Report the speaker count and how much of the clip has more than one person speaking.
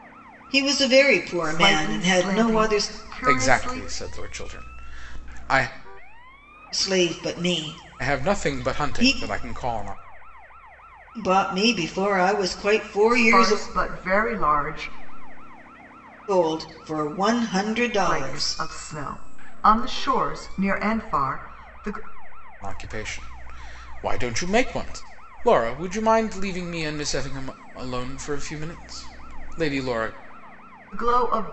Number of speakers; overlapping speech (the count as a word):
three, about 14%